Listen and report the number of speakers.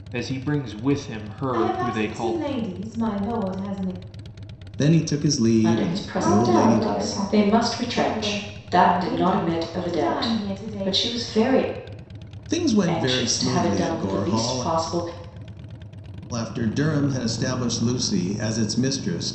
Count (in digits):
5